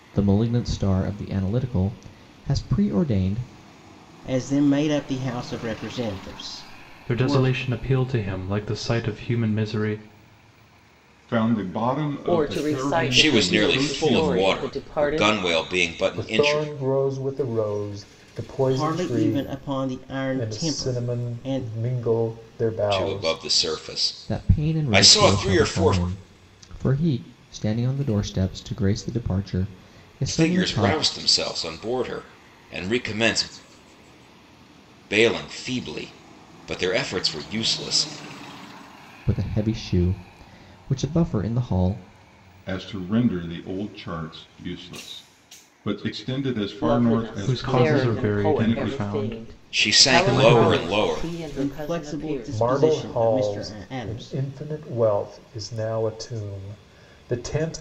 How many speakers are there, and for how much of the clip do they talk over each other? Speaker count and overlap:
7, about 29%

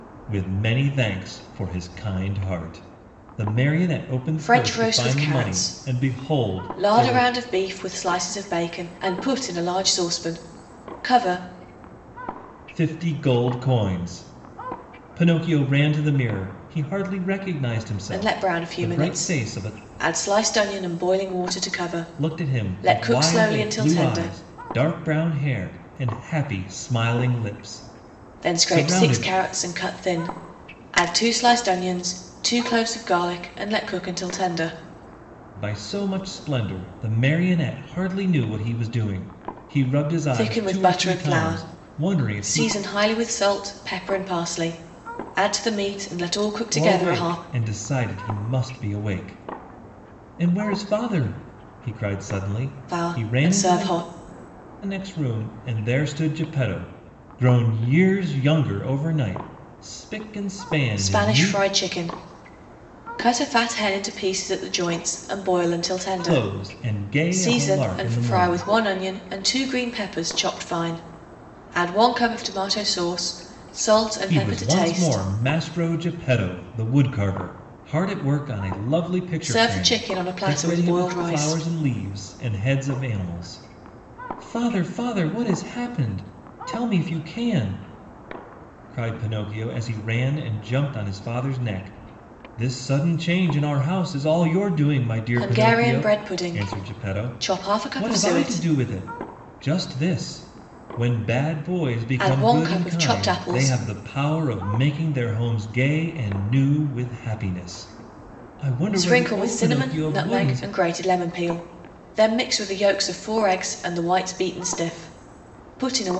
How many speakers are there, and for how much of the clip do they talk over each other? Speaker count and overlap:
2, about 21%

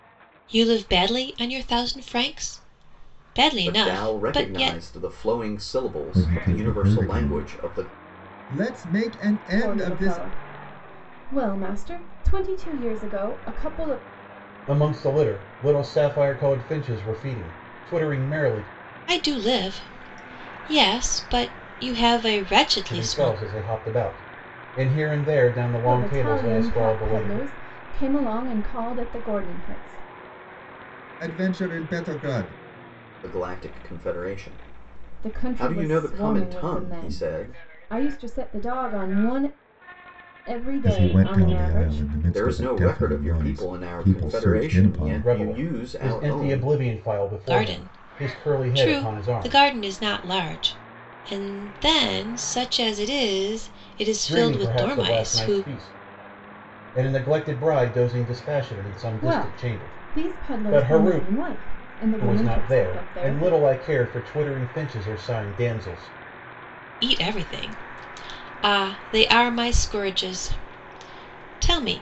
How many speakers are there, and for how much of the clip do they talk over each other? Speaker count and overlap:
5, about 29%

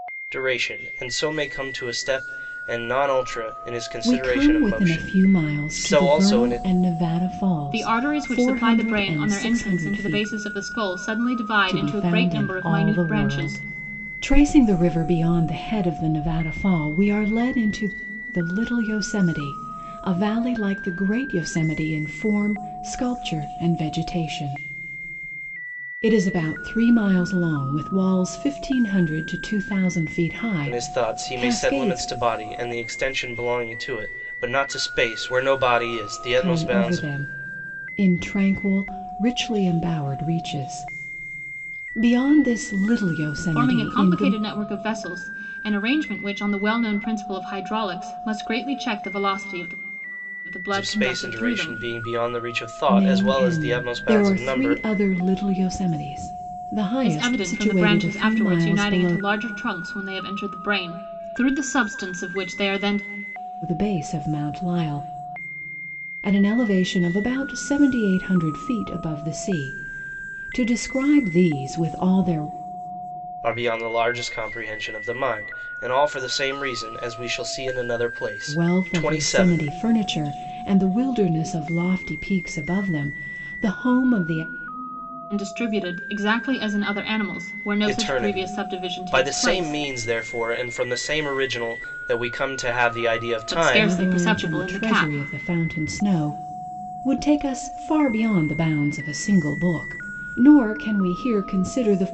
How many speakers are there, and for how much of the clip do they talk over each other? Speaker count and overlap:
3, about 20%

